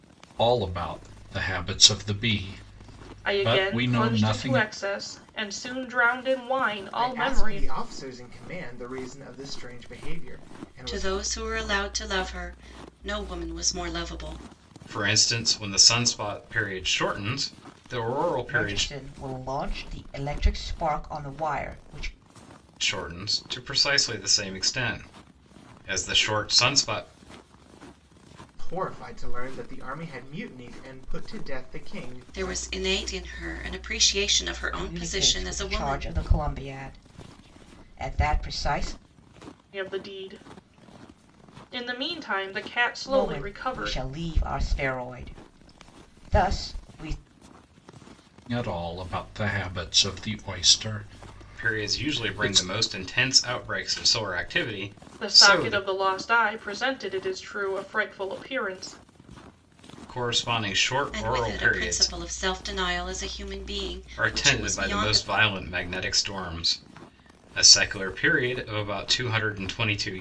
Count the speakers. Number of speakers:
six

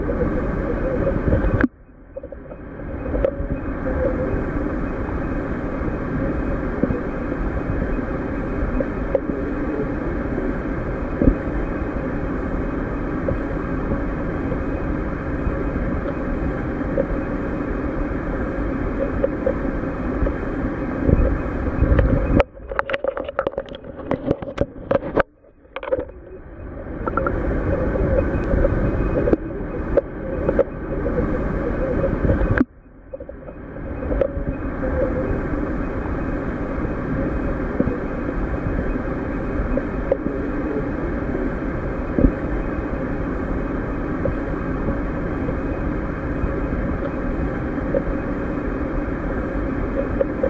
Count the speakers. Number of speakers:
zero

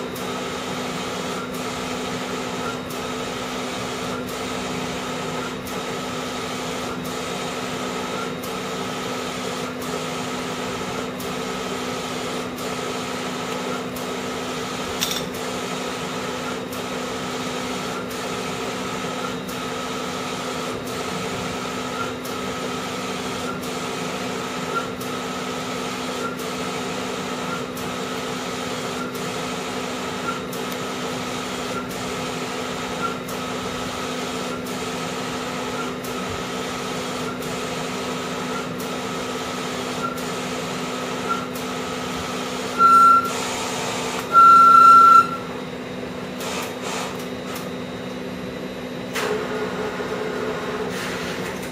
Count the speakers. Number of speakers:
zero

